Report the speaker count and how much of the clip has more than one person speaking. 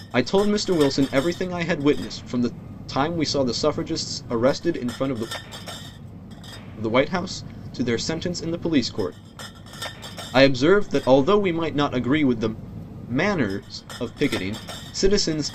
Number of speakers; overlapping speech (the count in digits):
1, no overlap